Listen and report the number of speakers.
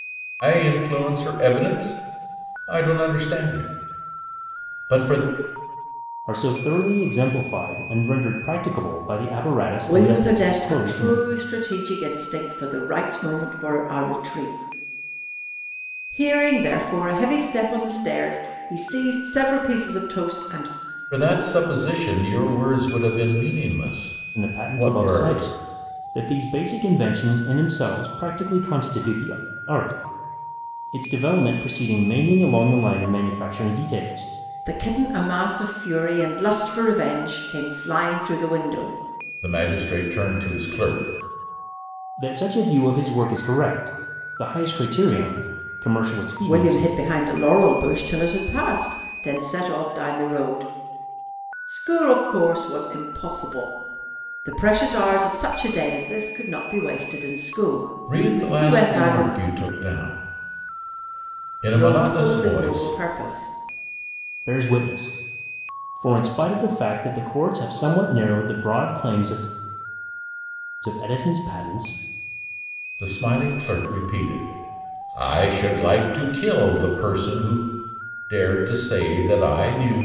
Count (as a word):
three